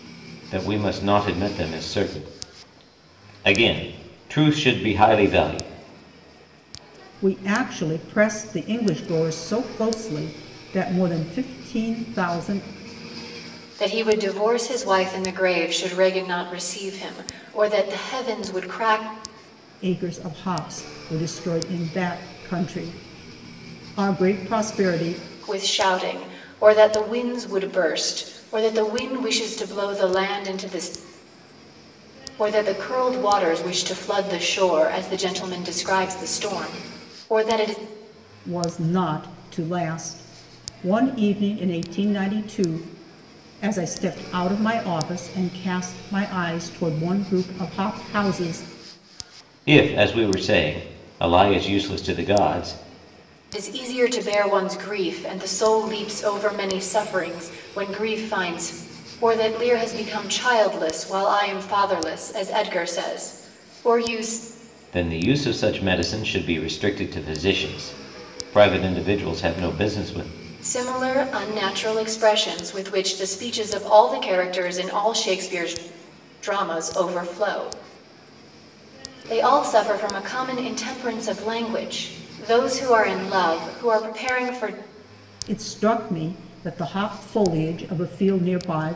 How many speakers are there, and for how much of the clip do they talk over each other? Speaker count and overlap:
three, no overlap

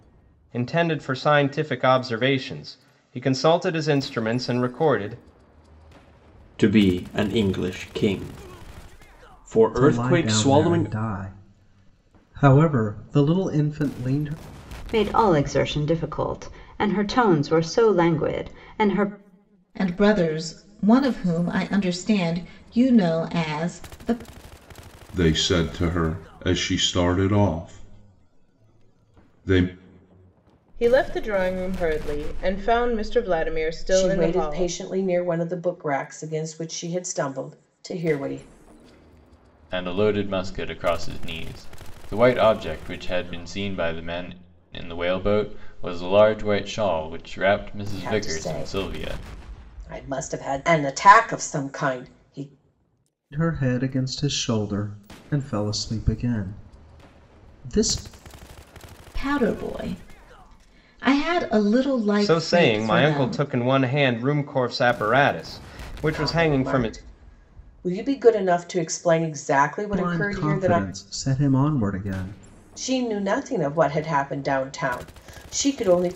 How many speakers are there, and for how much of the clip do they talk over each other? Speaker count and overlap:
nine, about 8%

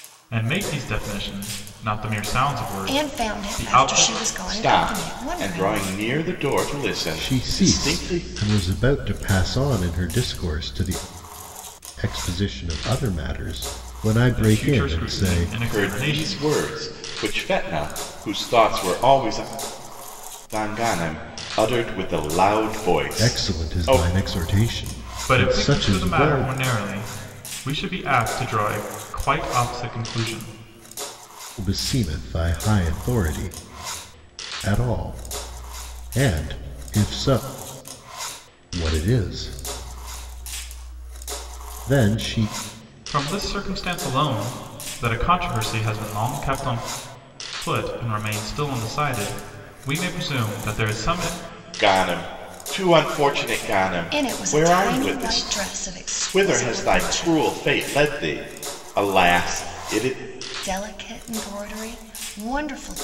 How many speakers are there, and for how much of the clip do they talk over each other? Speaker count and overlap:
four, about 17%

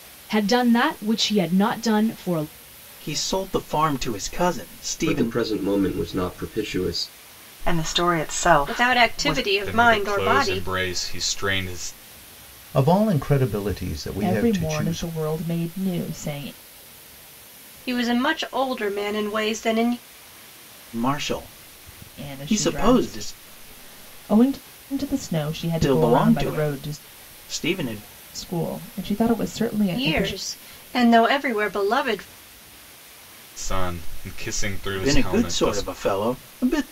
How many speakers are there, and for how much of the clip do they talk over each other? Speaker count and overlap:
eight, about 19%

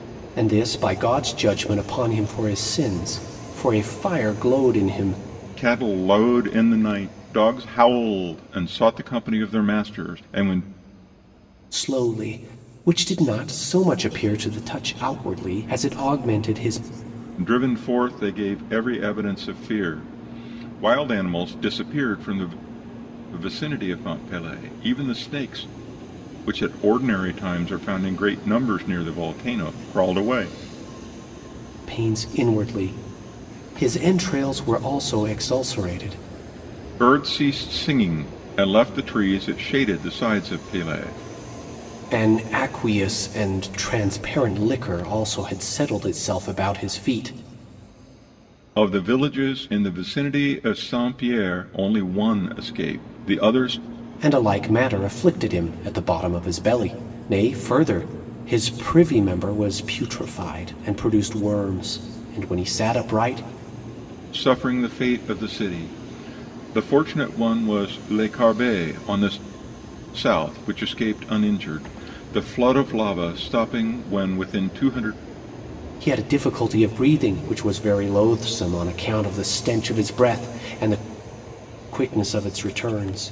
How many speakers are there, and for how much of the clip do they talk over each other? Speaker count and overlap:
two, no overlap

